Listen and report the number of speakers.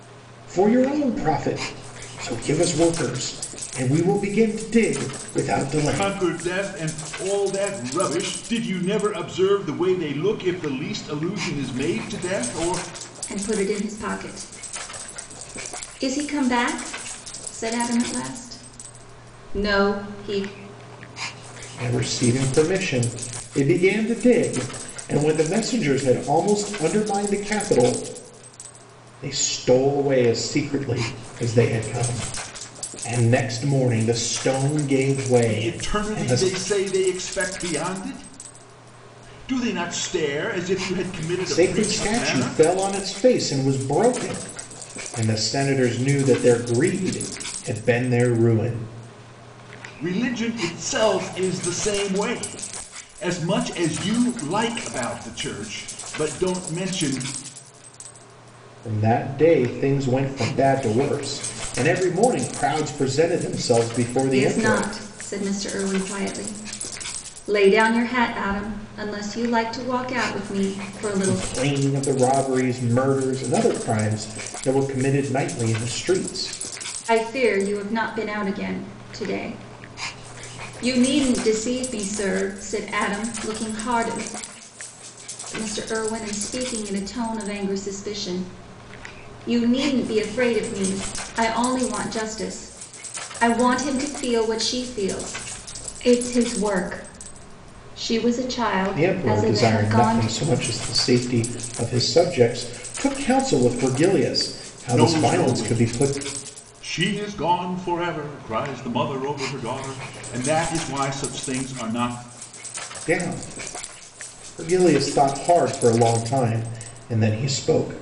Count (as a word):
three